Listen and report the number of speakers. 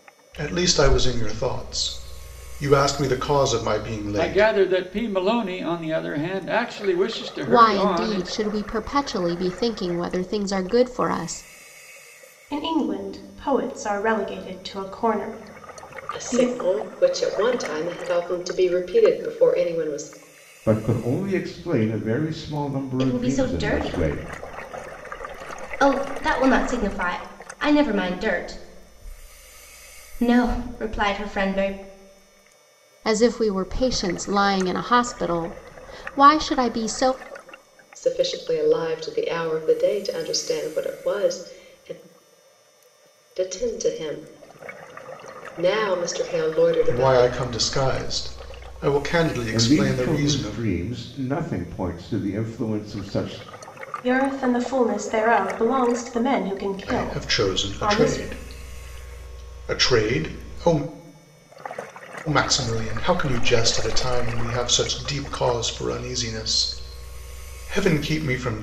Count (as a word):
seven